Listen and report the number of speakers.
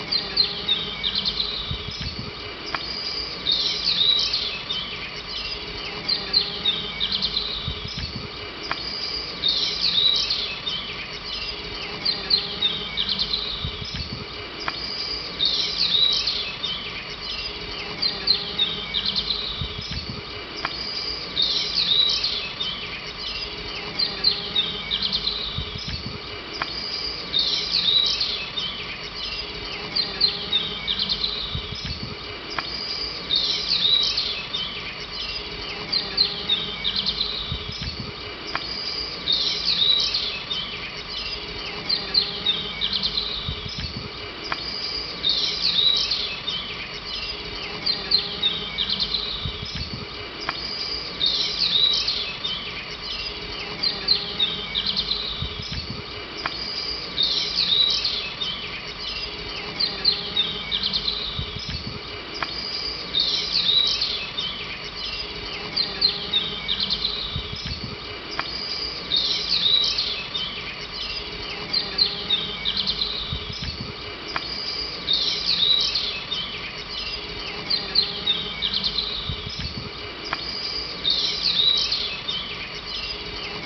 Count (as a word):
zero